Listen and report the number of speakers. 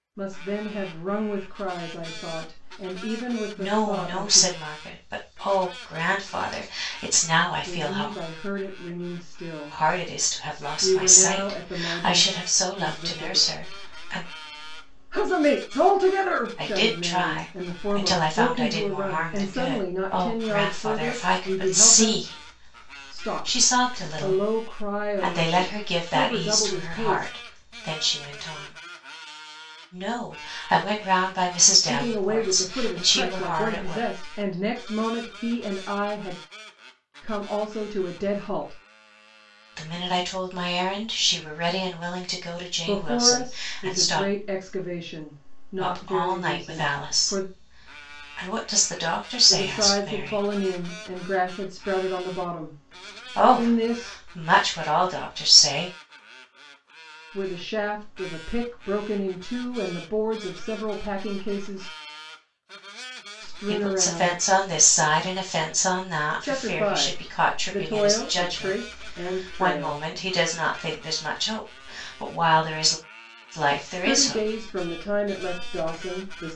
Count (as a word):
two